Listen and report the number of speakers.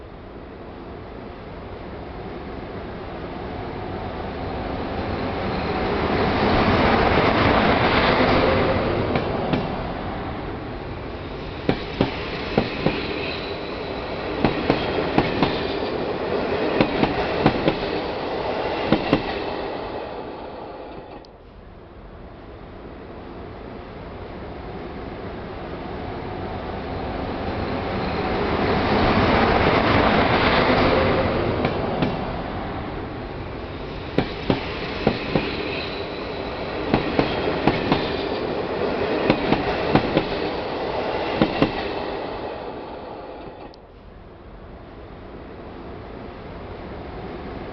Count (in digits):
0